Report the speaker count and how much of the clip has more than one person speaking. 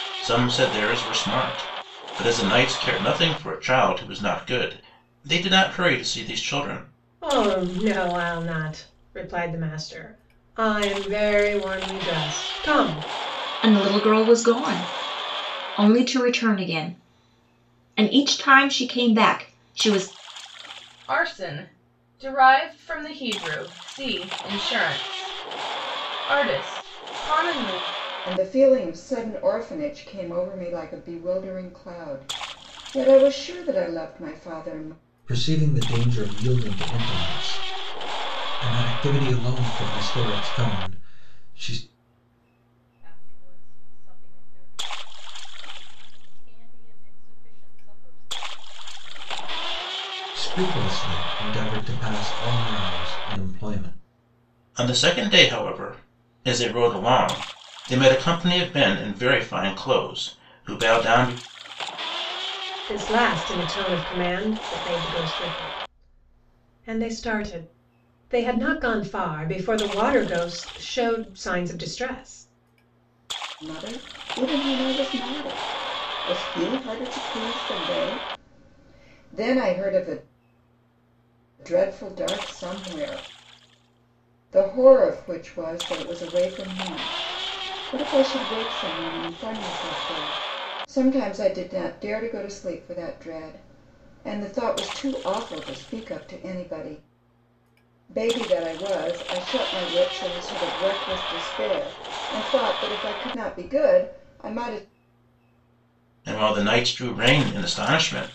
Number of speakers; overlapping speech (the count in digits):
7, no overlap